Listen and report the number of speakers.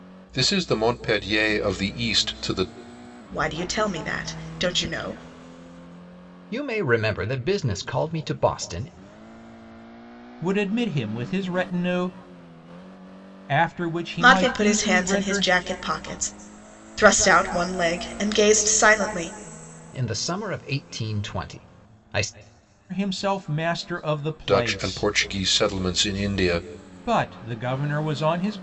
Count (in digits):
4